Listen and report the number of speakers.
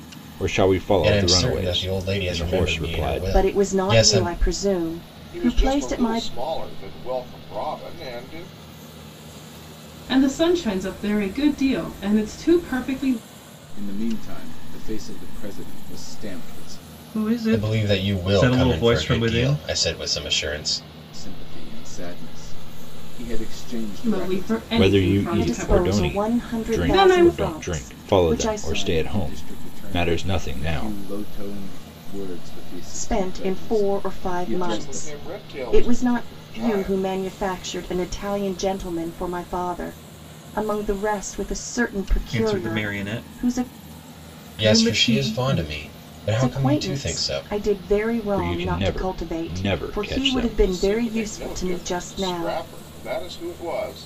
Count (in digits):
7